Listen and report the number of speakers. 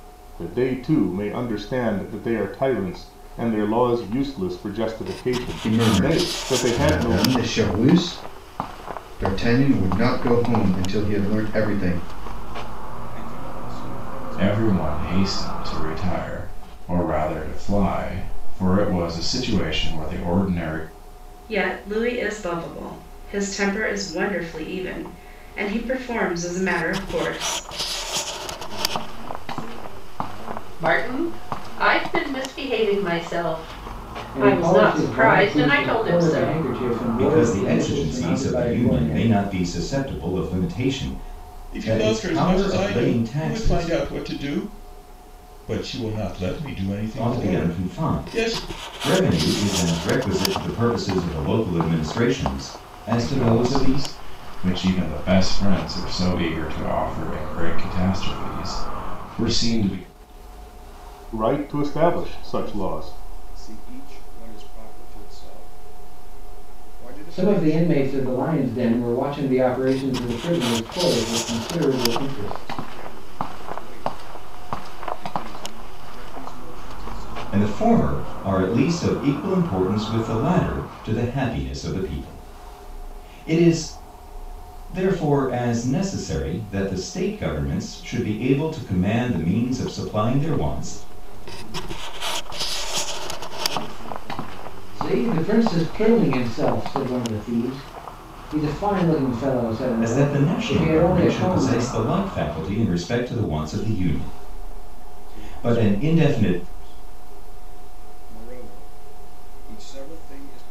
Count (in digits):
10